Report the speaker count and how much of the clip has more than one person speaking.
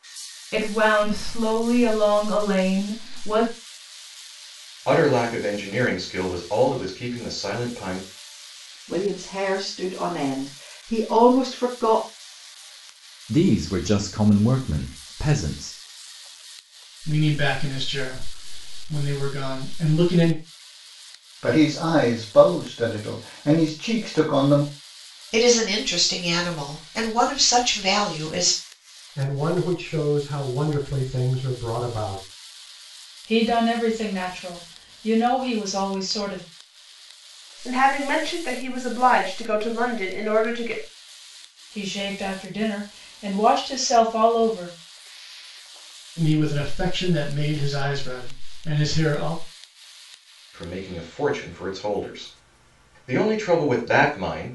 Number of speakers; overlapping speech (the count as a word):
ten, no overlap